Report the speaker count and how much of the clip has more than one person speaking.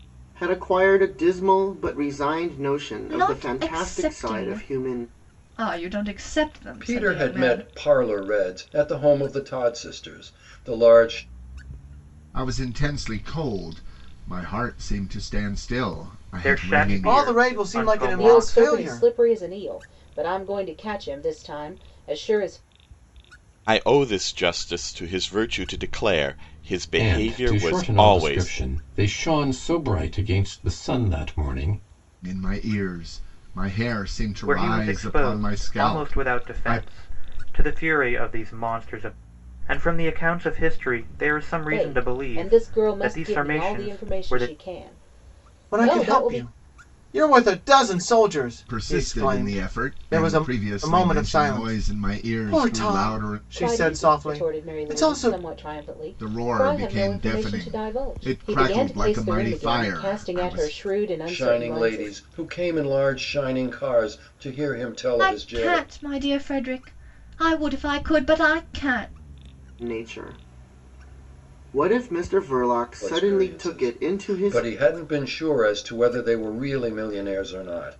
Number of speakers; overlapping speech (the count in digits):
9, about 35%